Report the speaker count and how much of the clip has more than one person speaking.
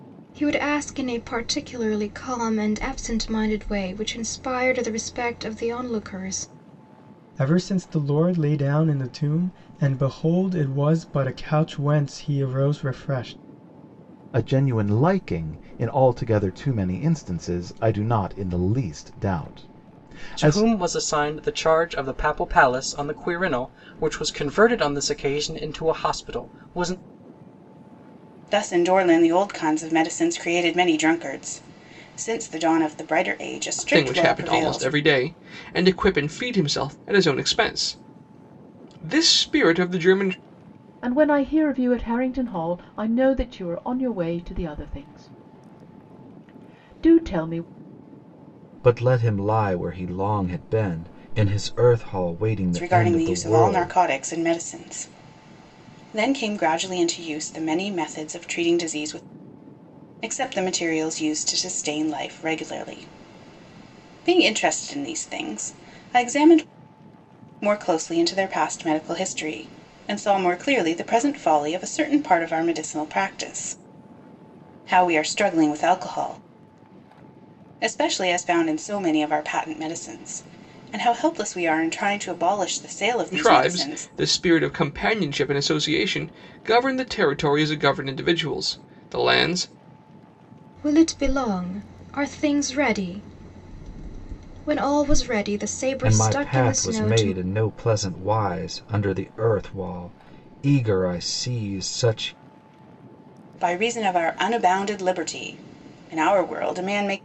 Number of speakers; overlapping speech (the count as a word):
eight, about 5%